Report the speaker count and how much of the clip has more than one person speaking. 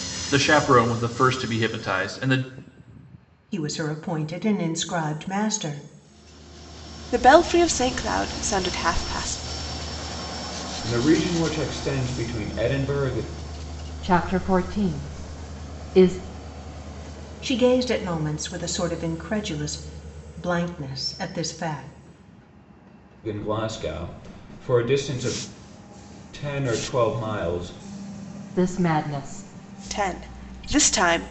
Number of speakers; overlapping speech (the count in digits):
5, no overlap